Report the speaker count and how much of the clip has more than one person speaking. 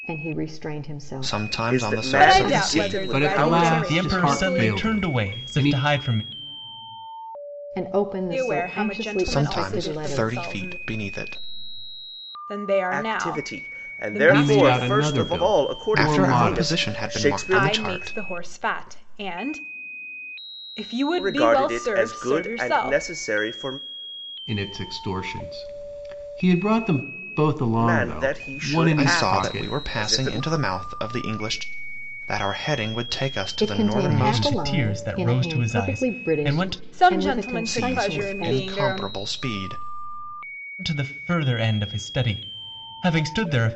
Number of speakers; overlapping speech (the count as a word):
six, about 51%